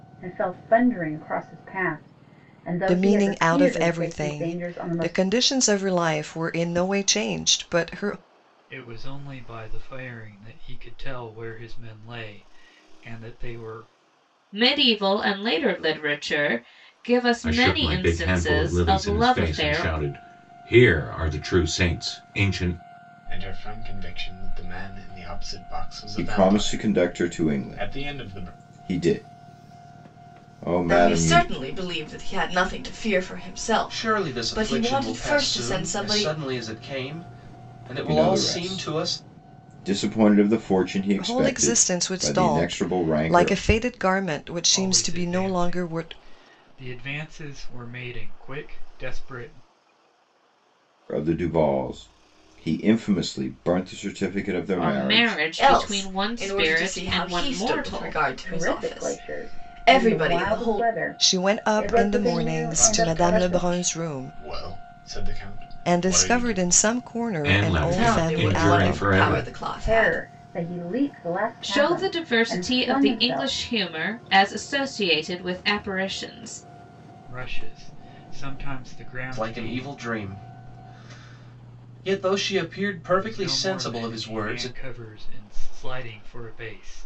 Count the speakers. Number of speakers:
9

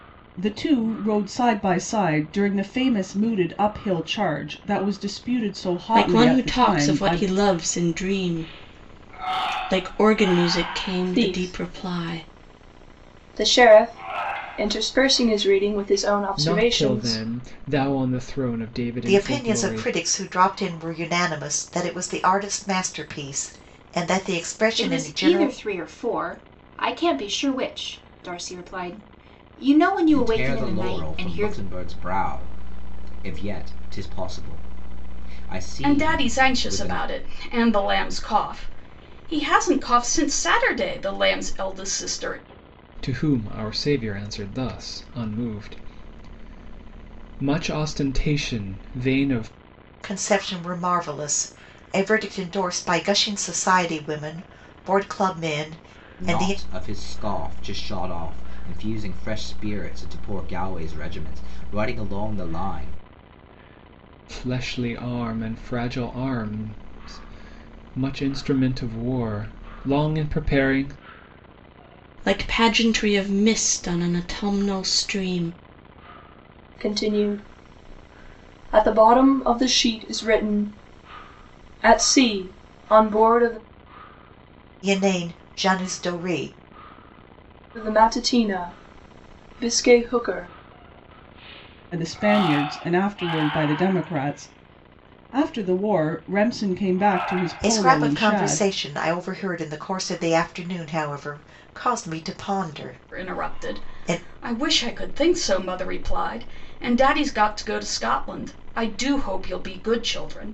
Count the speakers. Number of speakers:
8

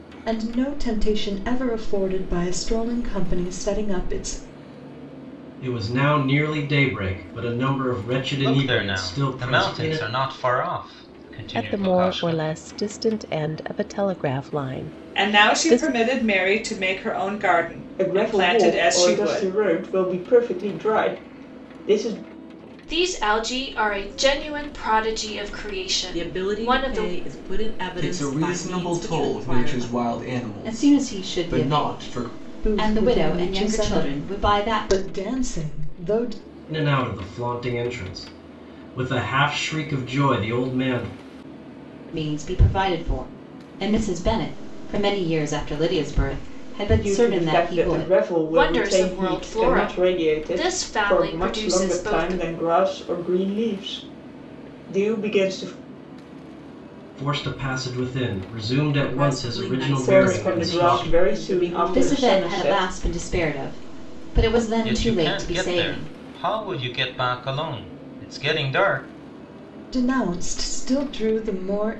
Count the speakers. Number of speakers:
10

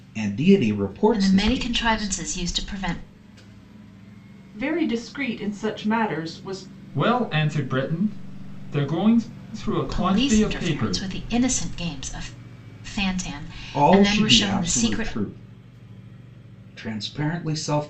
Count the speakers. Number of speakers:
4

